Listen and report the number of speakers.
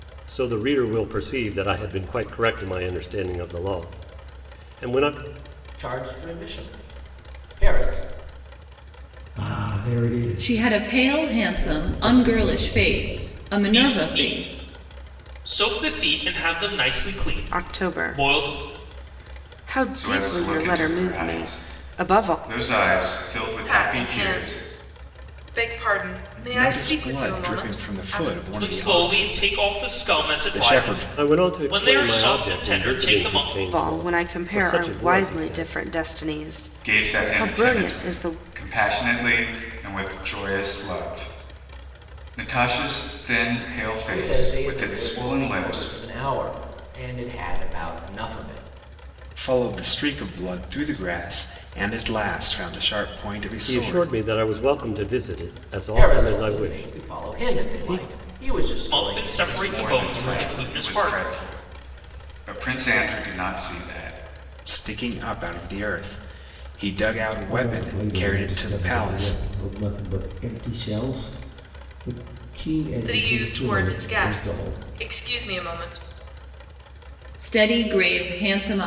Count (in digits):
9